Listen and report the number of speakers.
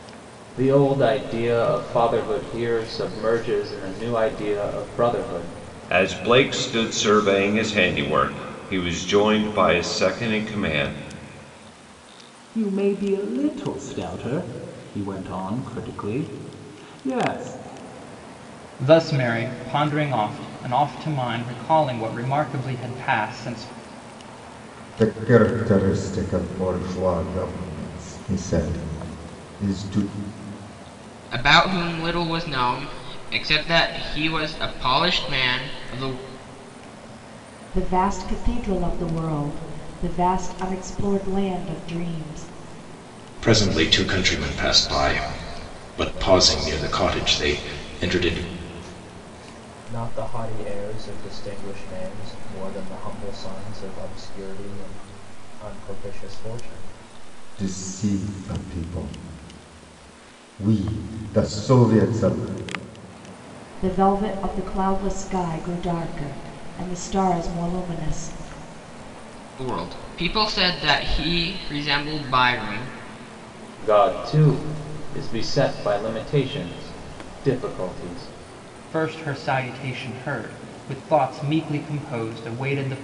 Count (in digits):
9